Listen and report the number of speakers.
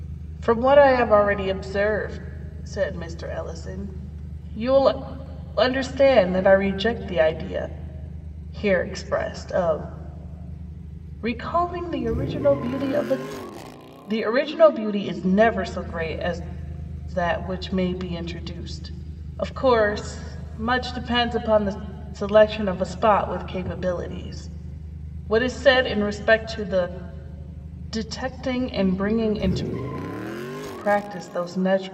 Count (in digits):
1